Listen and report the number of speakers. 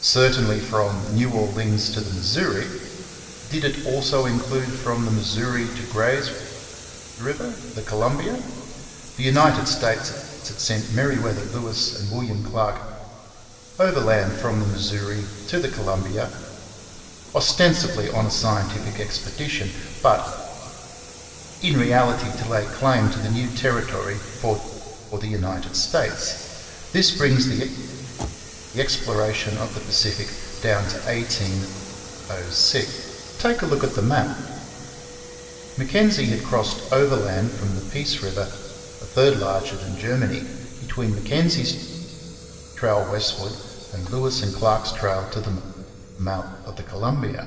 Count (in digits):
1